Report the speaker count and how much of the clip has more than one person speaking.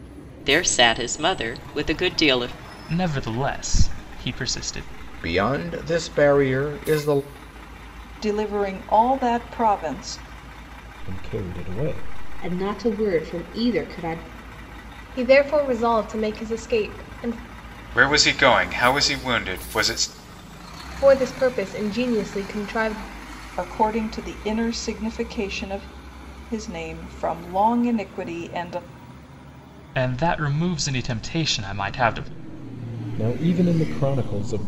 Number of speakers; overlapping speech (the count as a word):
eight, no overlap